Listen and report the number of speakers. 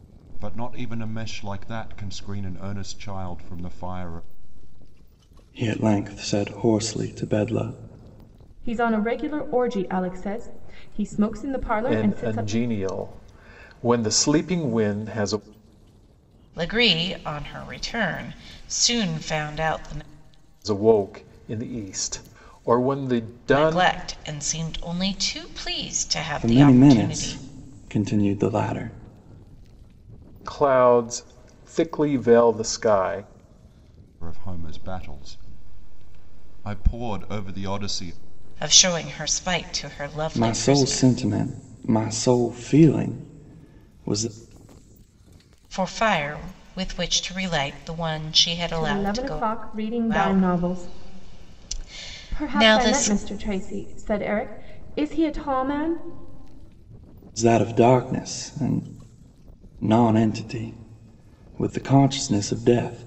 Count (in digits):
5